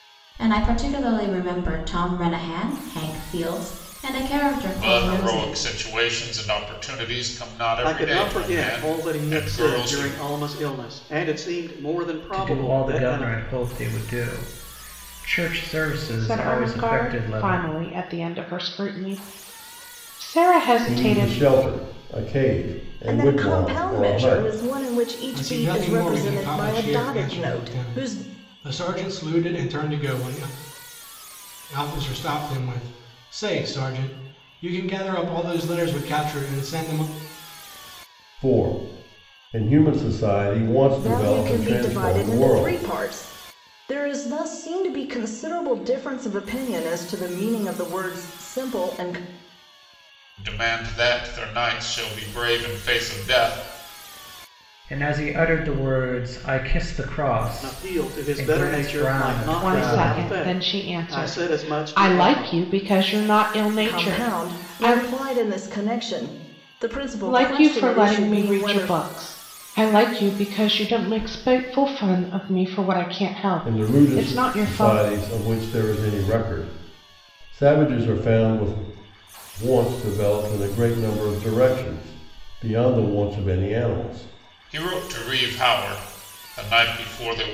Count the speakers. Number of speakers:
eight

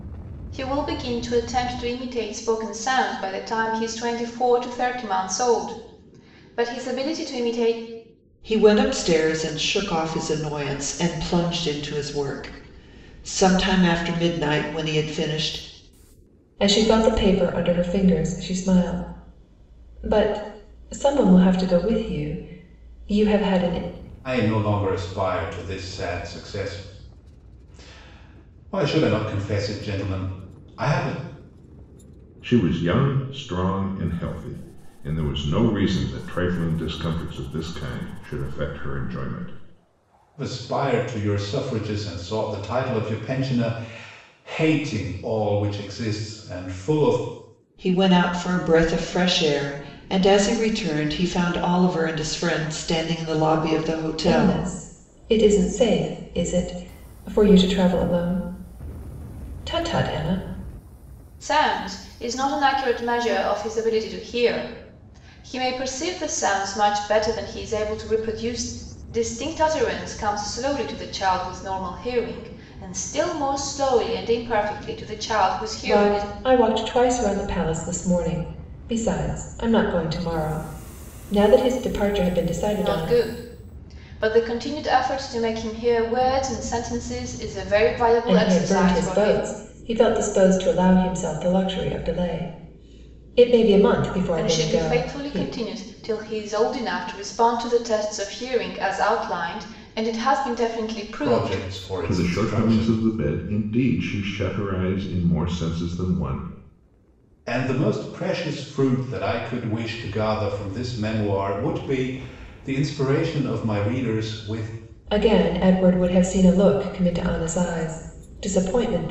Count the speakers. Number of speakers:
five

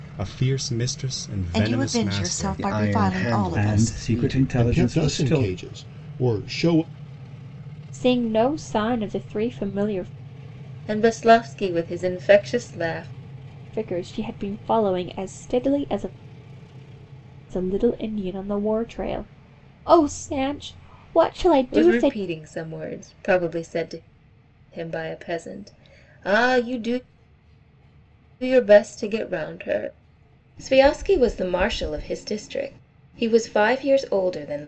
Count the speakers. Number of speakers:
seven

